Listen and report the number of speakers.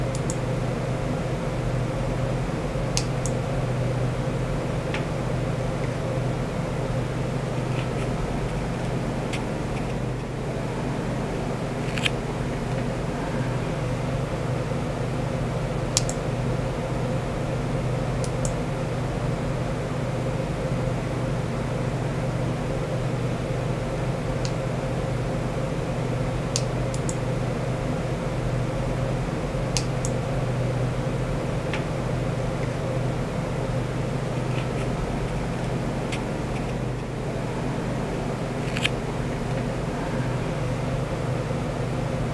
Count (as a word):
zero